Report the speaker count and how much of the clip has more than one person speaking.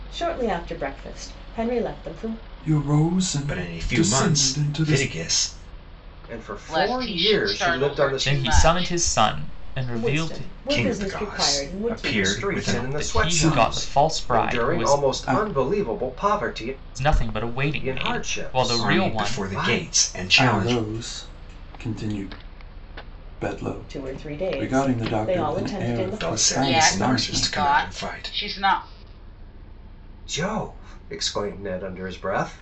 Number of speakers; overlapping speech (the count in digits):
6, about 50%